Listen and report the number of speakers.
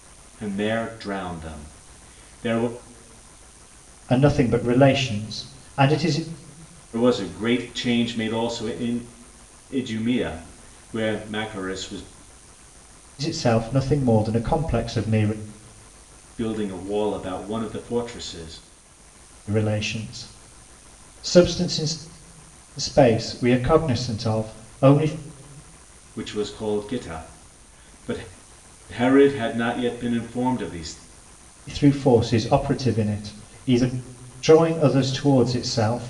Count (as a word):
two